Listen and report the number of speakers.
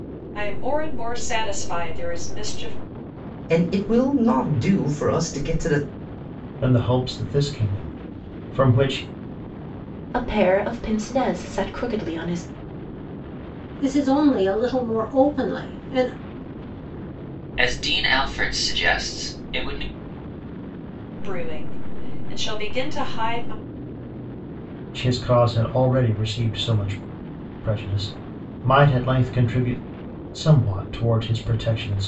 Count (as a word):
six